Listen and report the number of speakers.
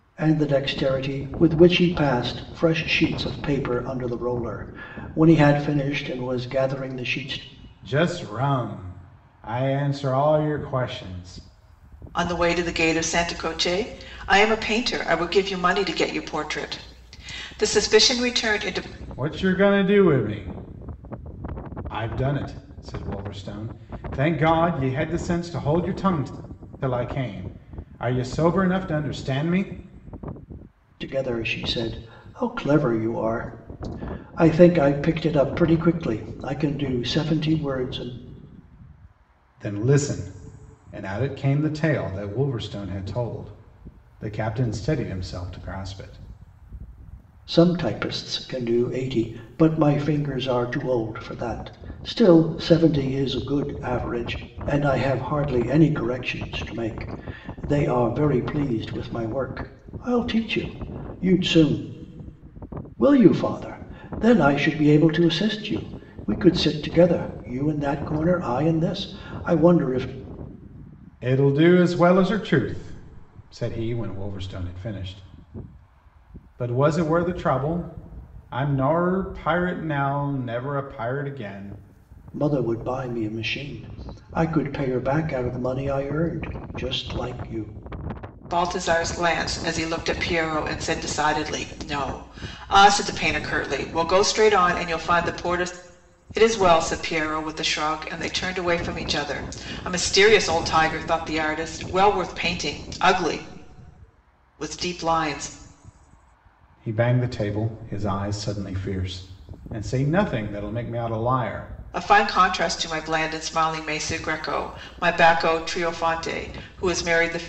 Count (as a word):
three